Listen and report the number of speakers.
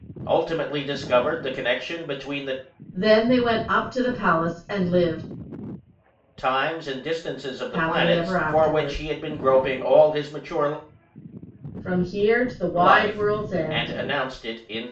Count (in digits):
2